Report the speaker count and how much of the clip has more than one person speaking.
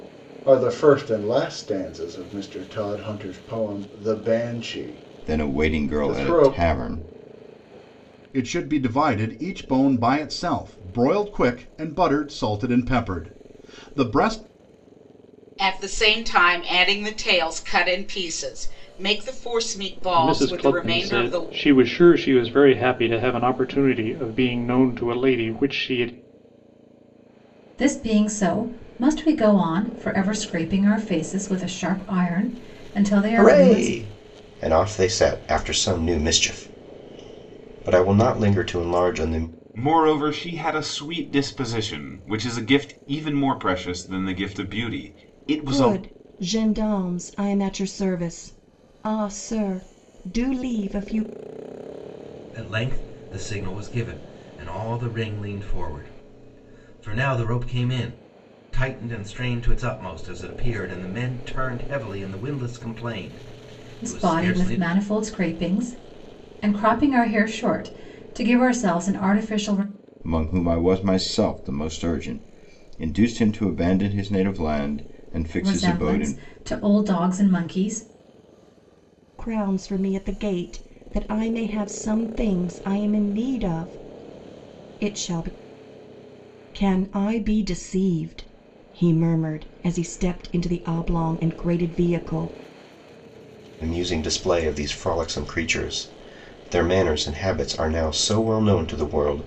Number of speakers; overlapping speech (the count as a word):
ten, about 5%